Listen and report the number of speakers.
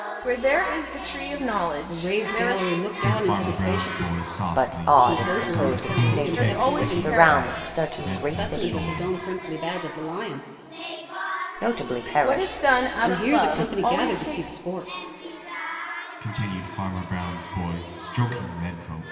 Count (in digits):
4